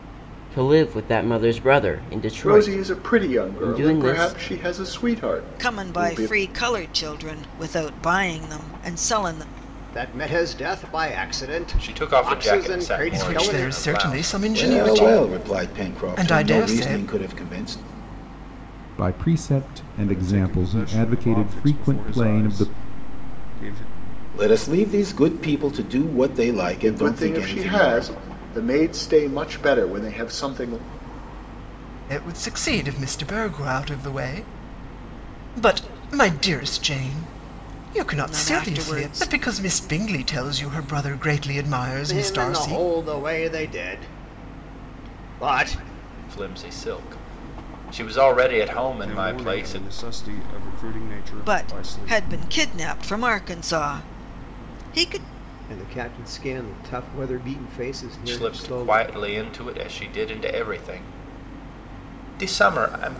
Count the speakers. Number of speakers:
nine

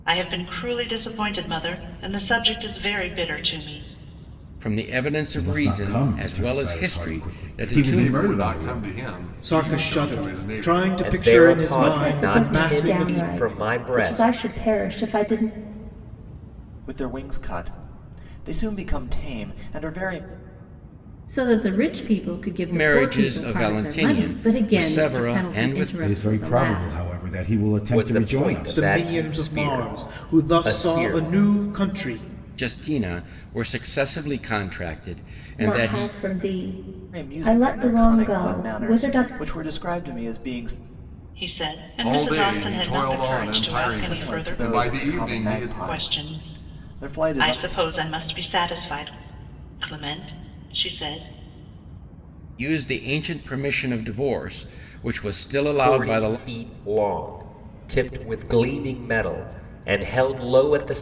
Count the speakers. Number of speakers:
nine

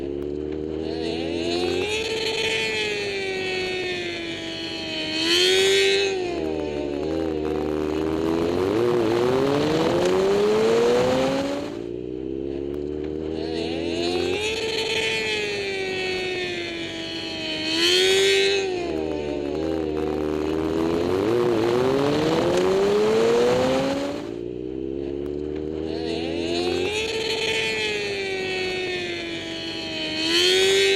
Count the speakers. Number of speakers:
zero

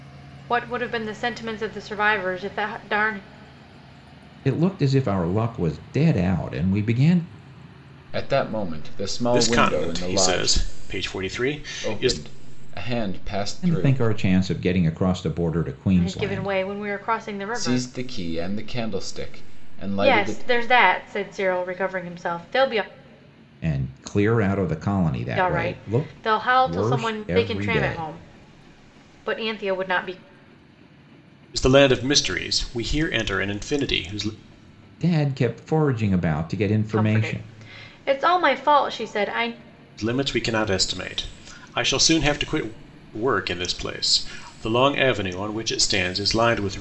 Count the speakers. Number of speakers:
four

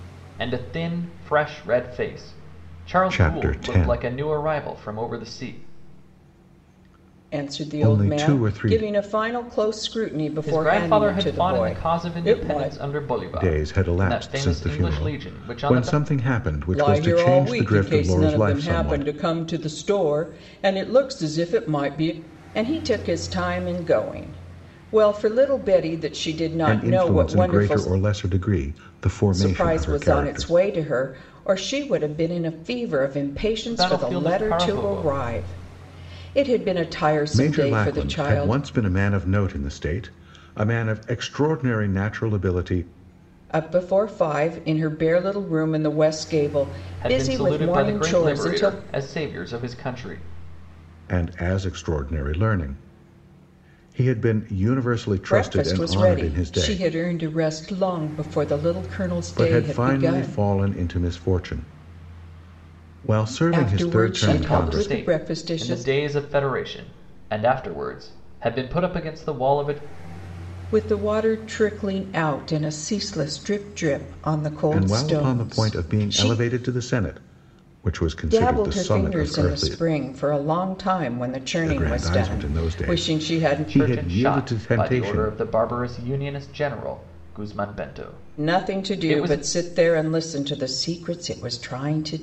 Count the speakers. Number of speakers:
three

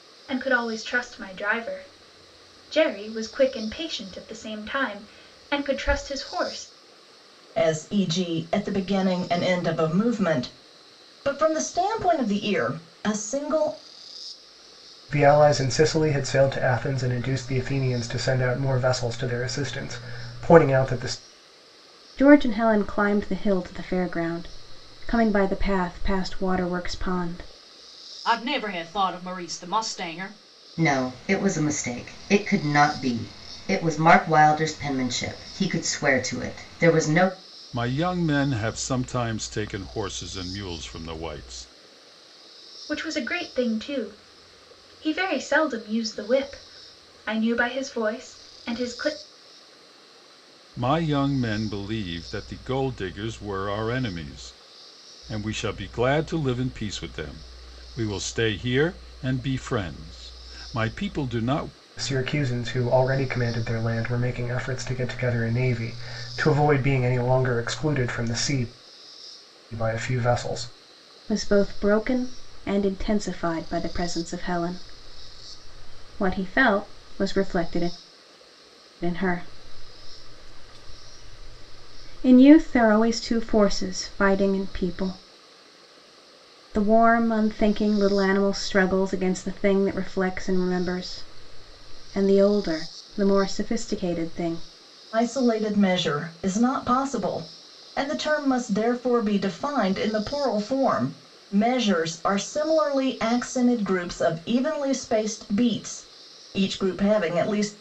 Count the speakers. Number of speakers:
seven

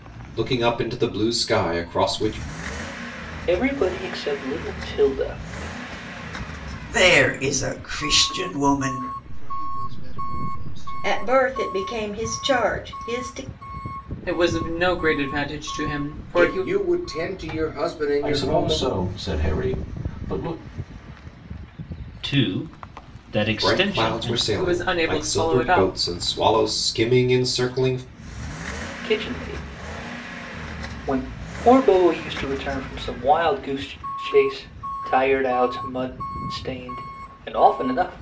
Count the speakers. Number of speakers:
nine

